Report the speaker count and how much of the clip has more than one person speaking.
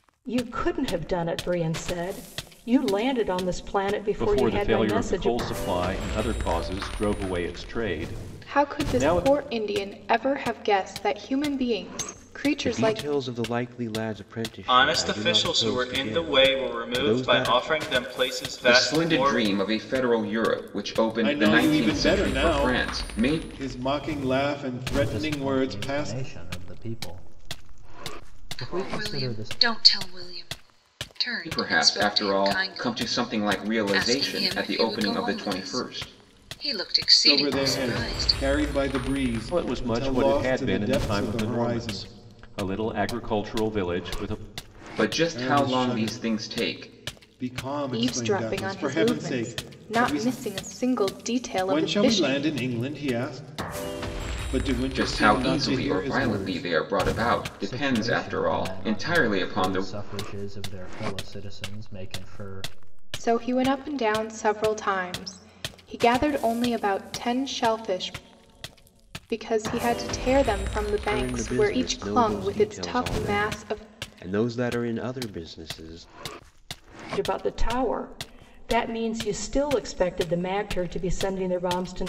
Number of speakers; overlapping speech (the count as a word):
nine, about 37%